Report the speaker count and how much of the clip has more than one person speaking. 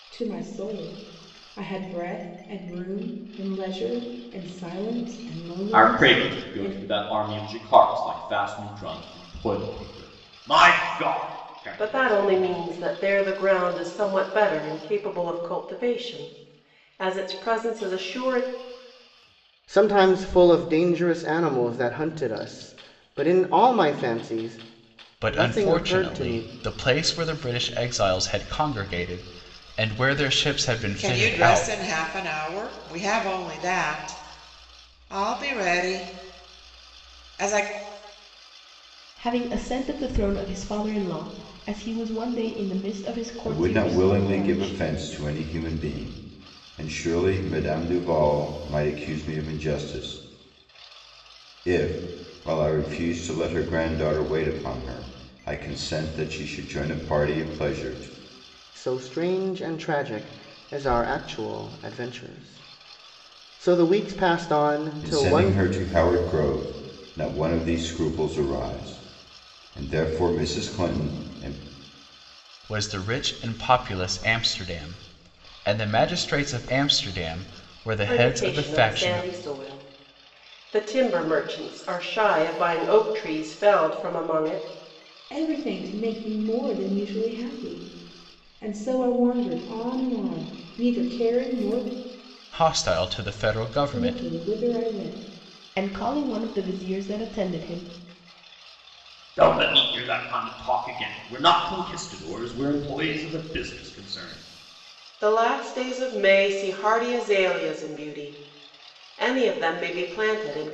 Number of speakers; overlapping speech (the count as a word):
eight, about 7%